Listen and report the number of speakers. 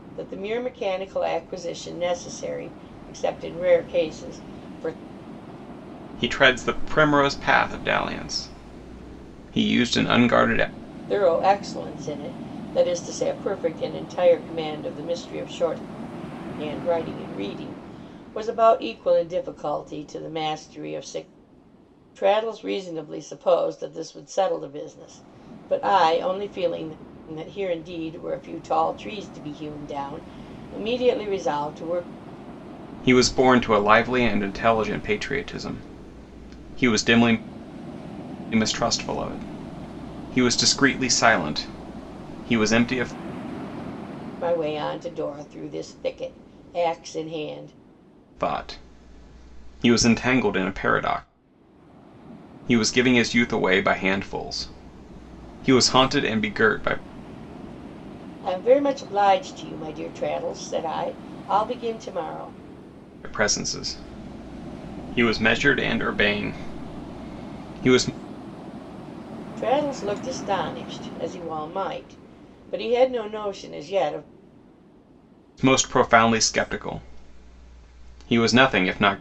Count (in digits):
2